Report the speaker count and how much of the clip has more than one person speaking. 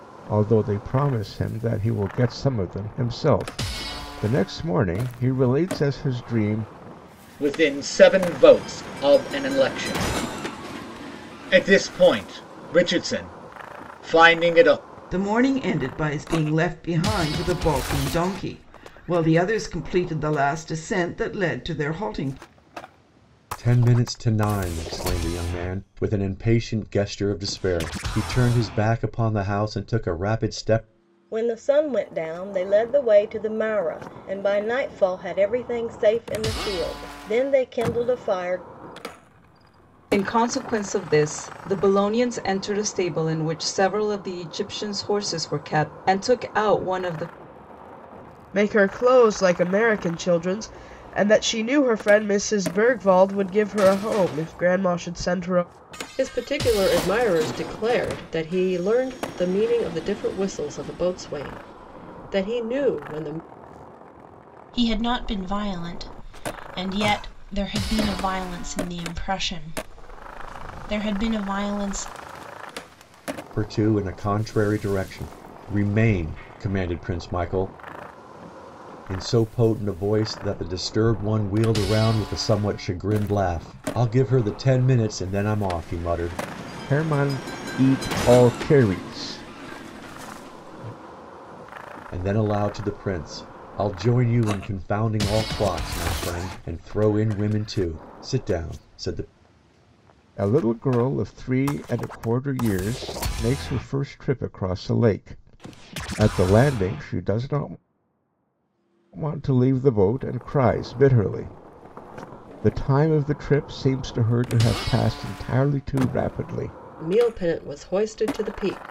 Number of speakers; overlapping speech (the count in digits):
9, no overlap